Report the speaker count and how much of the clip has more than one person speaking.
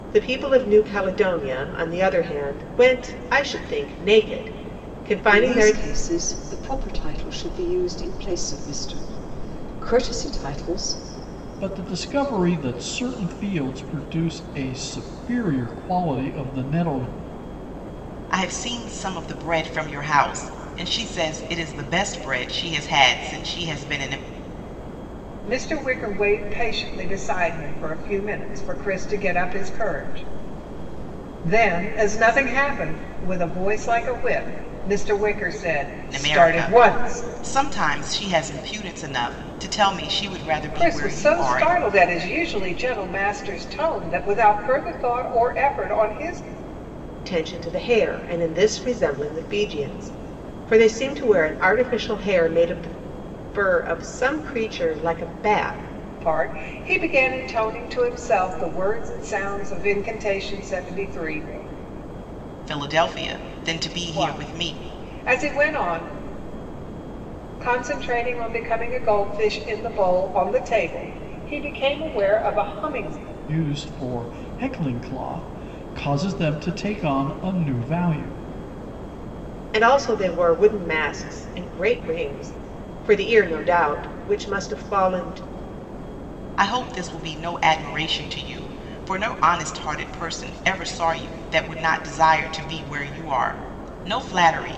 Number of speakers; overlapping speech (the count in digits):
5, about 4%